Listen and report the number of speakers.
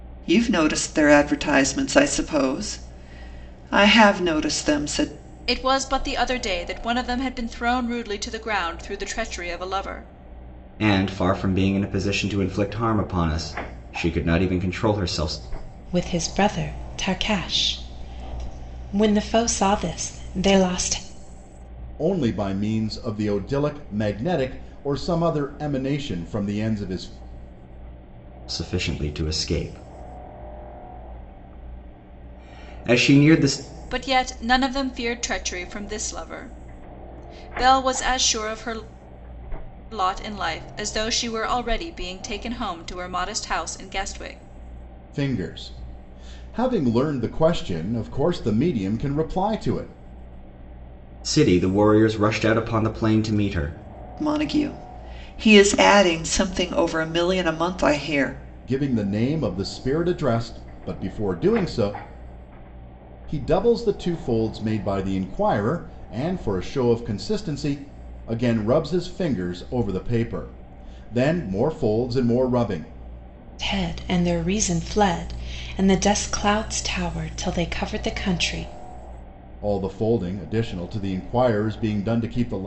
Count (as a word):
five